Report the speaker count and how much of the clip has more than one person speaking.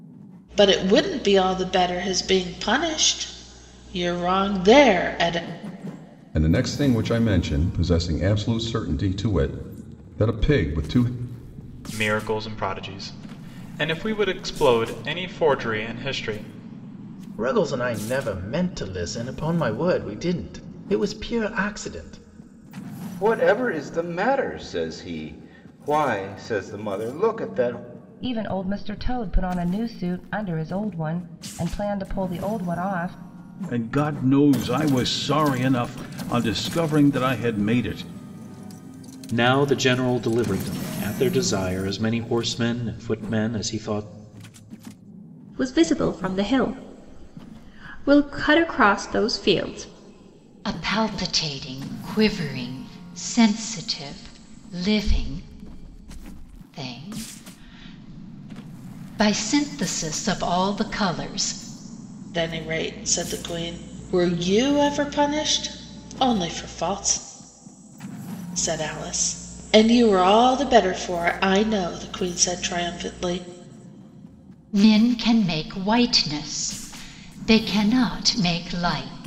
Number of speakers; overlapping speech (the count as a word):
ten, no overlap